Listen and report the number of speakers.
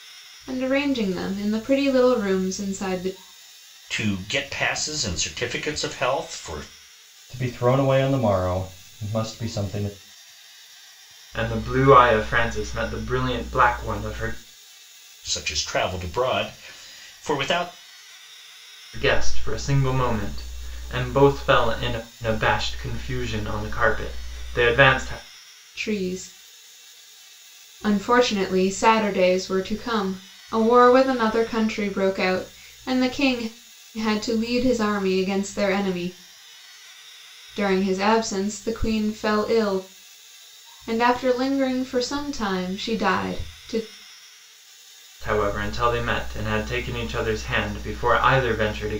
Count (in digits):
4